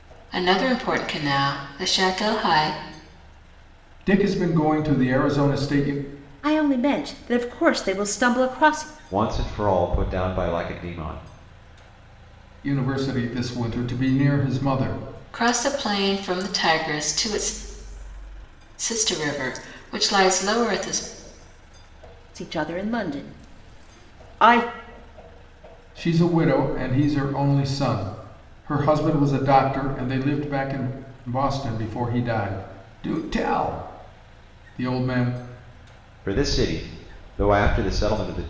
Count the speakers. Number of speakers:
four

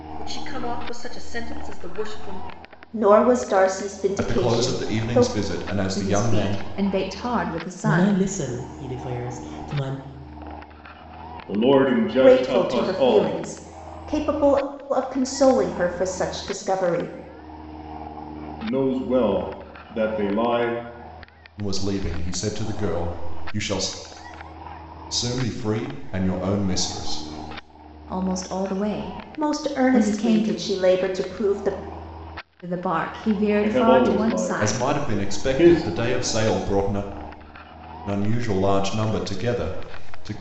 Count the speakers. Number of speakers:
six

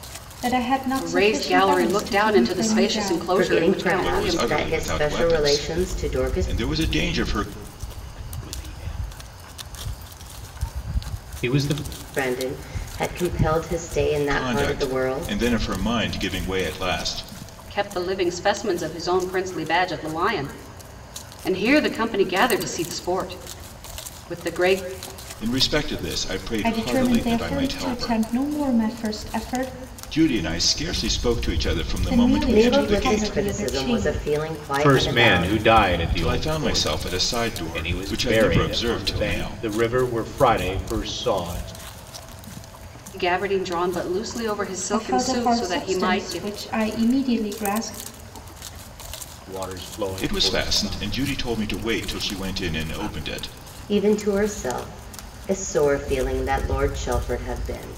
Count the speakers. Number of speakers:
five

